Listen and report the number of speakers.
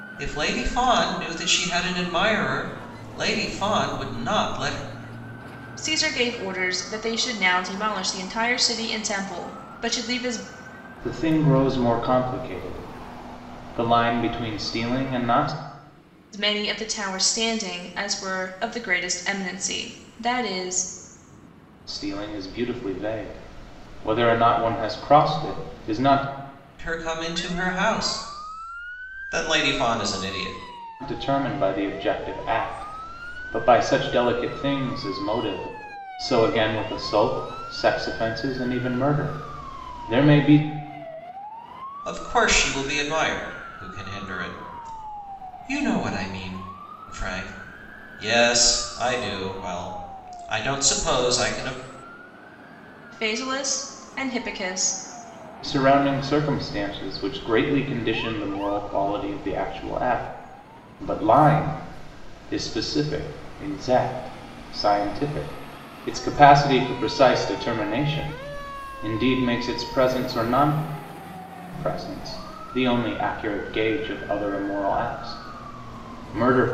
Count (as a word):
three